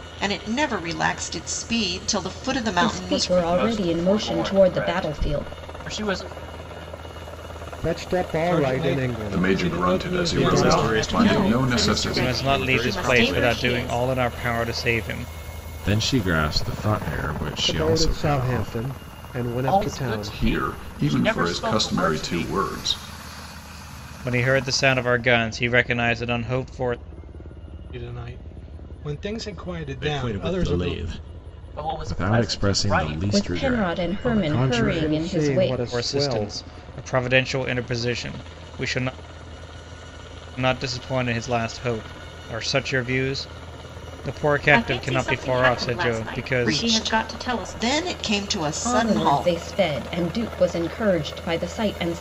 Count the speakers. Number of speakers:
10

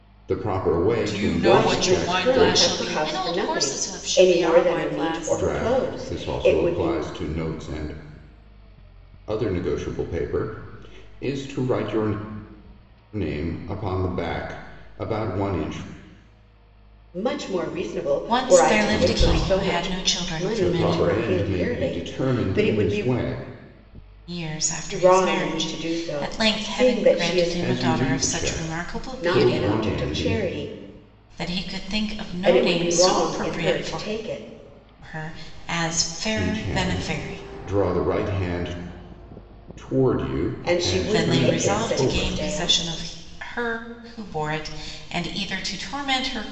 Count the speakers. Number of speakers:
3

